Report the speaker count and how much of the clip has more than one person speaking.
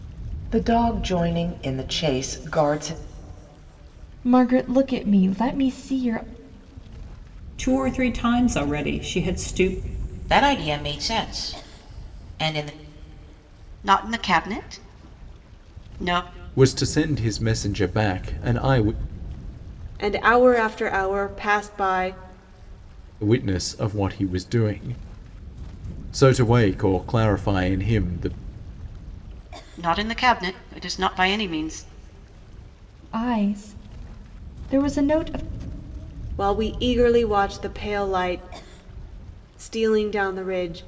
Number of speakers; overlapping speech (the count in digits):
7, no overlap